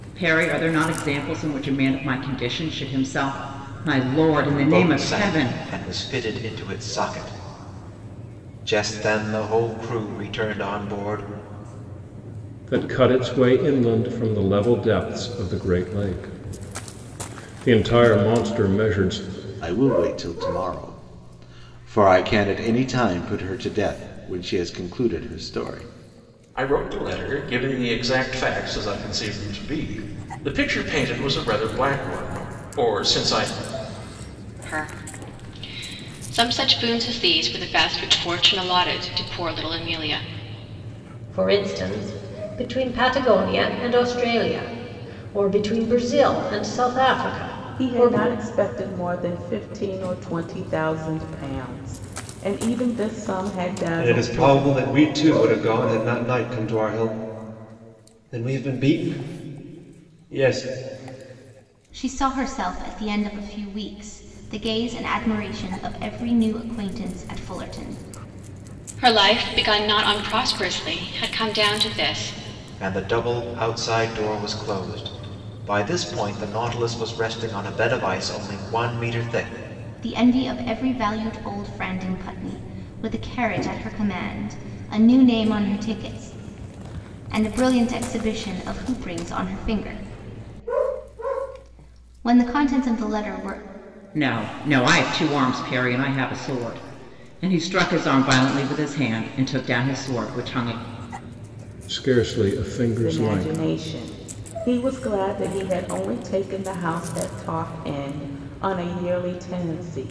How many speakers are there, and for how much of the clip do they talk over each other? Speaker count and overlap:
ten, about 3%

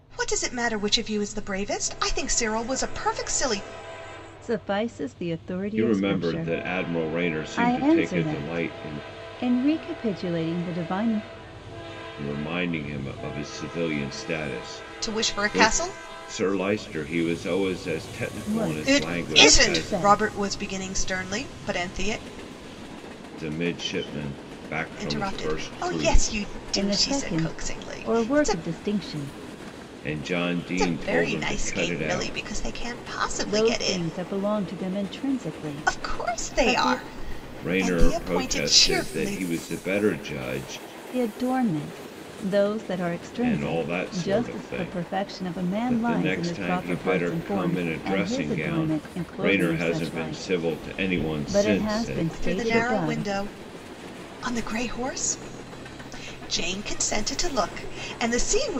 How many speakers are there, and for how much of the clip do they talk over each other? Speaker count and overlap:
three, about 38%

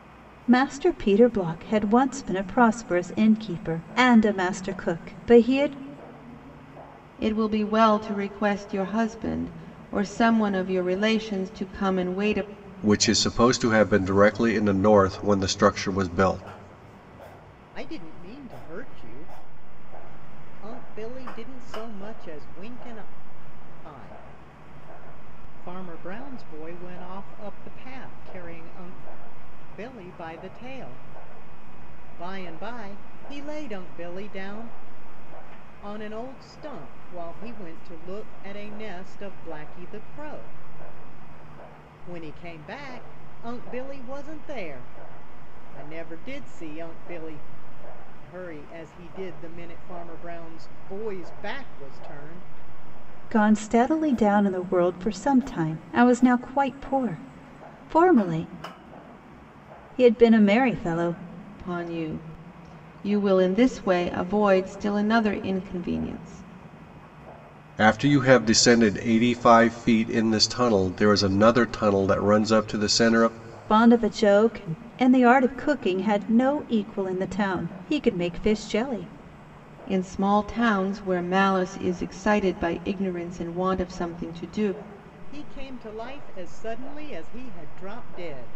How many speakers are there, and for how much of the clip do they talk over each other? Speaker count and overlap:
four, no overlap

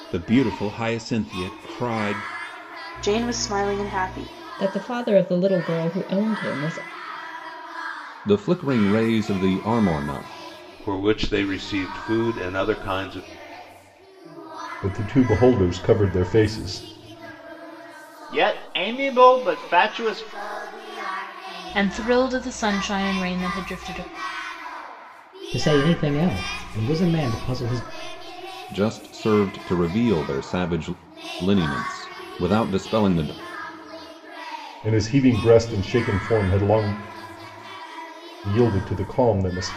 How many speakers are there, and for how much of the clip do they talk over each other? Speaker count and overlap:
nine, no overlap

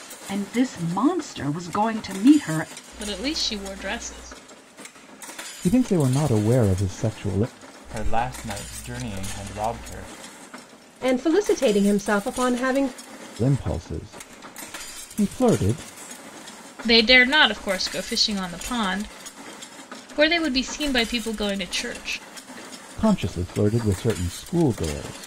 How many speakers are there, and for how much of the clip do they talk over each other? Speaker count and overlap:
five, no overlap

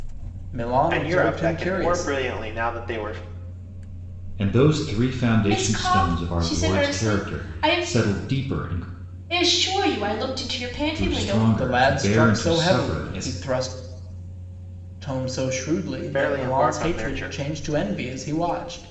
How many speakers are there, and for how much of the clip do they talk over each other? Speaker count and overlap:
four, about 41%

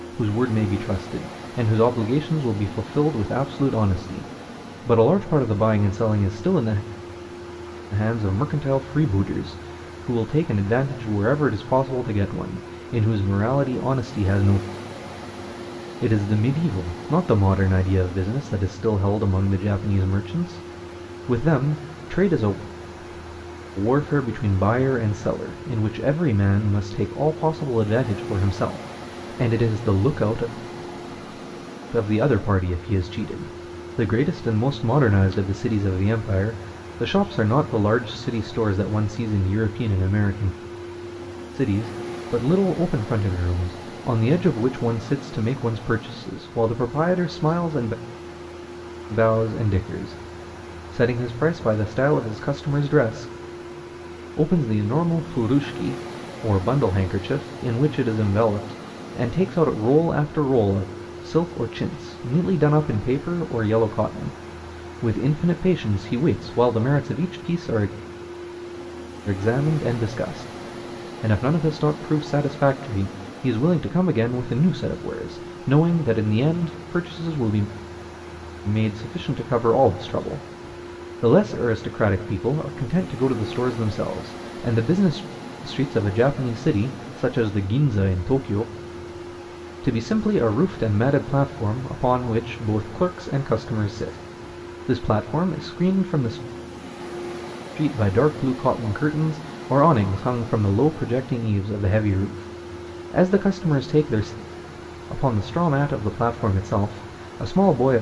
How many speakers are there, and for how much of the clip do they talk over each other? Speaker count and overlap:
one, no overlap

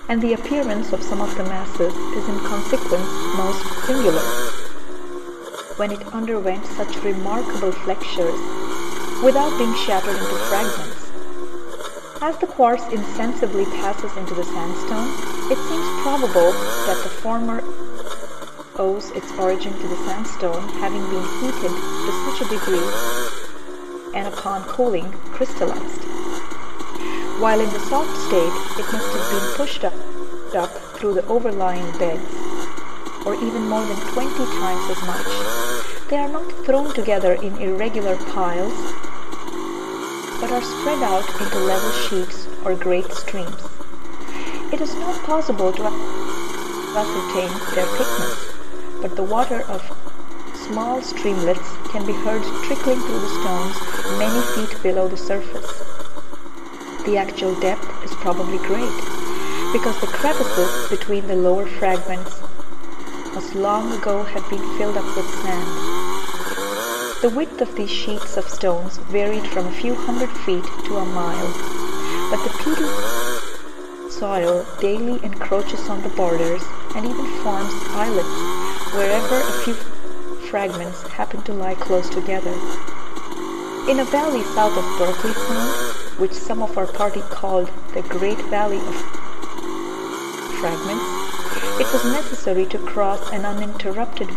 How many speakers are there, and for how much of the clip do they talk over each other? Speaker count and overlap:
one, no overlap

